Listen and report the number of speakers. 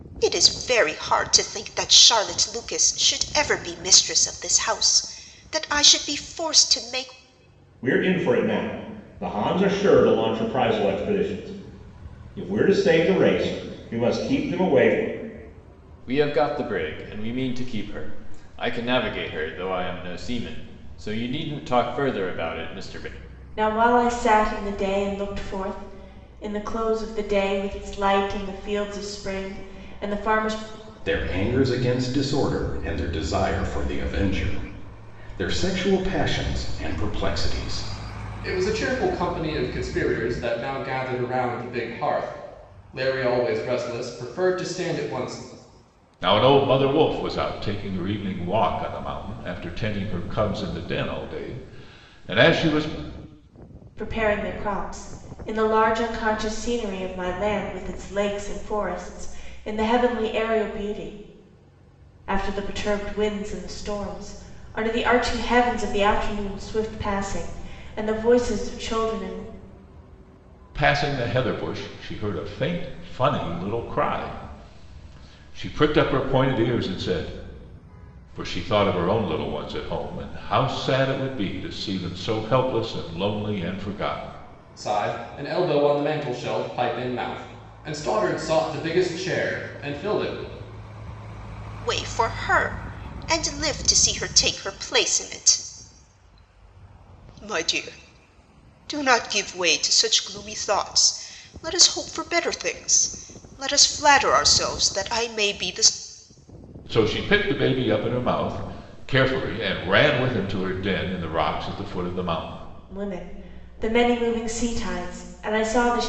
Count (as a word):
seven